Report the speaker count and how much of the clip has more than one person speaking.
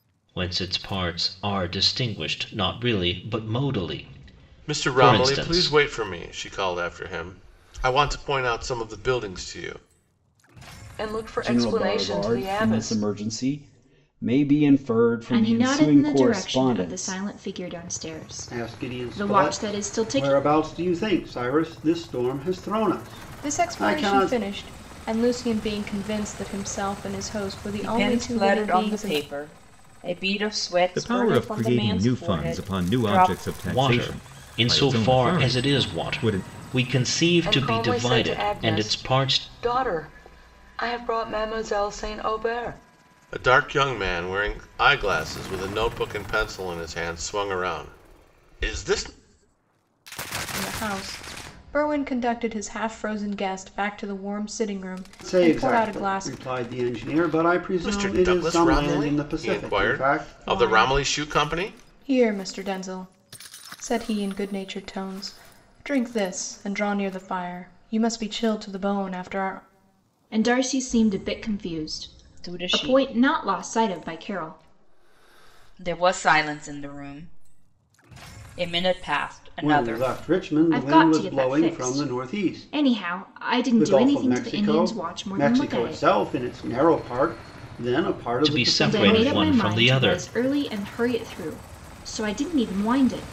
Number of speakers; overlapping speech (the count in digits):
9, about 33%